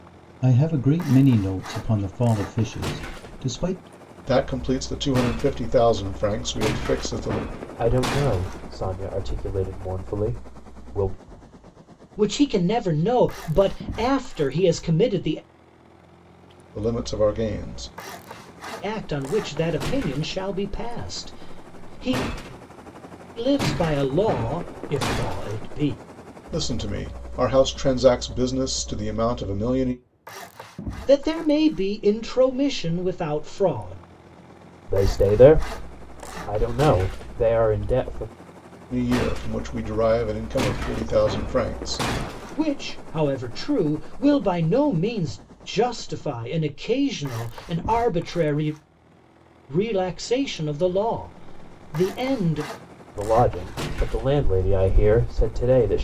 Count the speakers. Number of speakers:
4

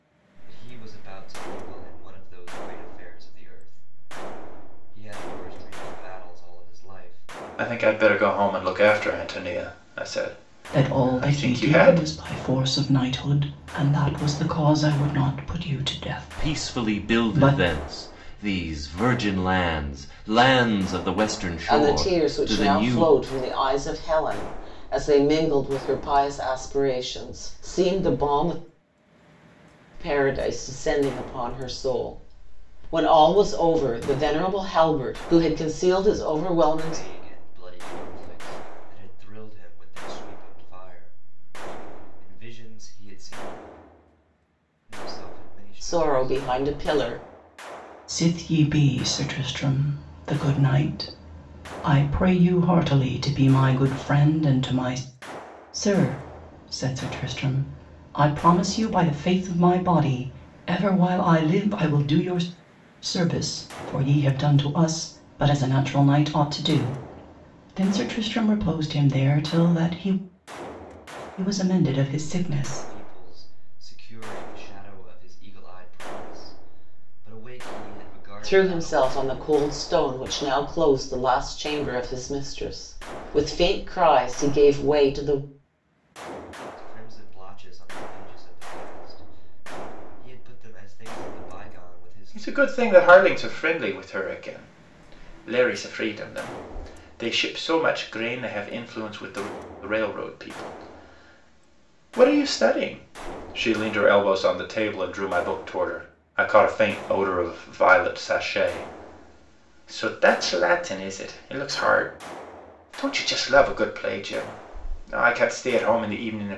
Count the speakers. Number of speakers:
5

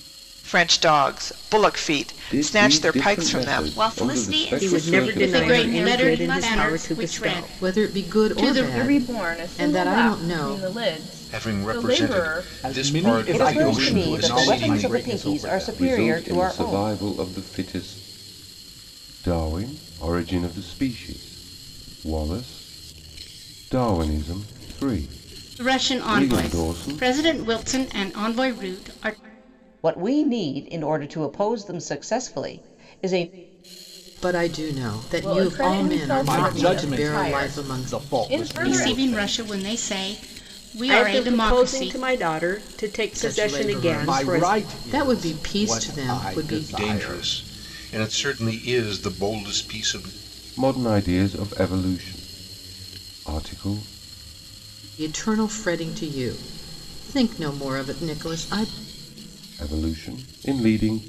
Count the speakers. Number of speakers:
10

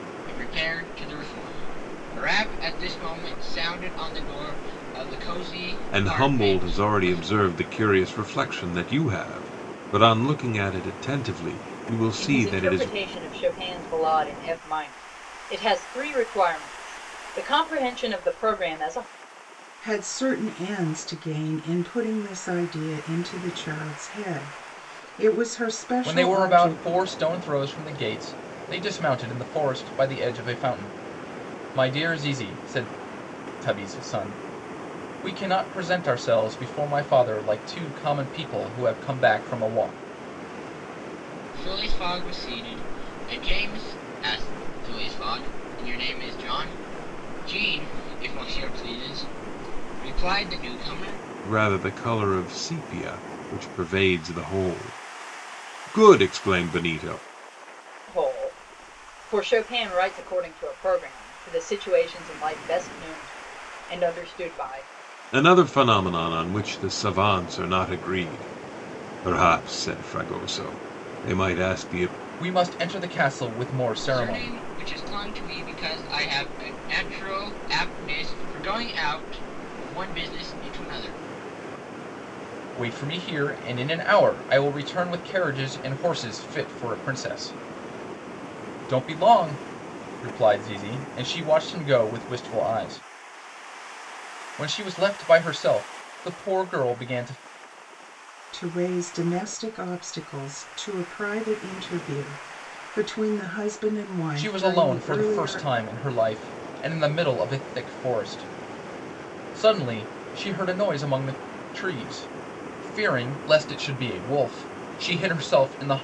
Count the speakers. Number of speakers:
5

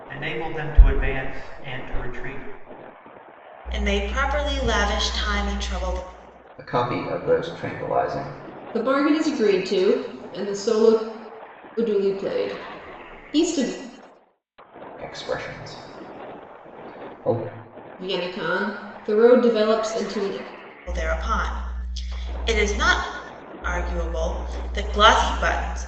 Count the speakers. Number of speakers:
4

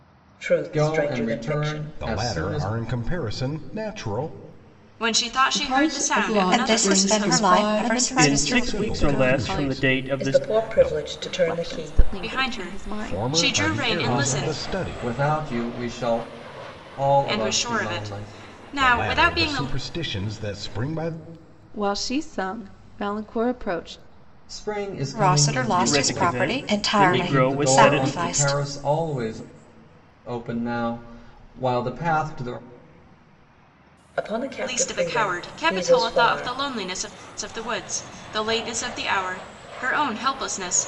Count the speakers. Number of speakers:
8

